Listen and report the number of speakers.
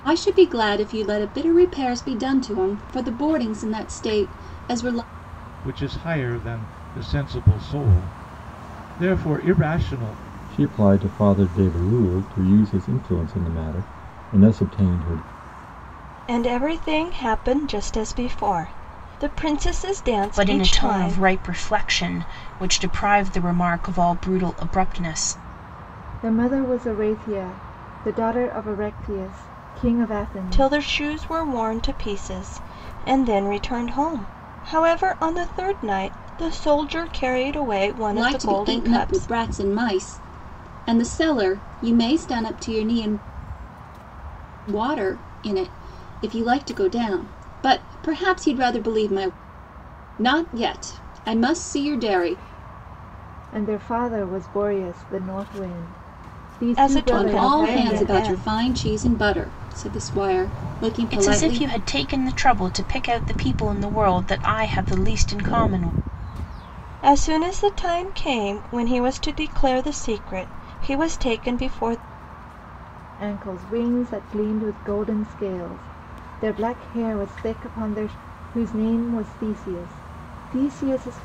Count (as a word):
six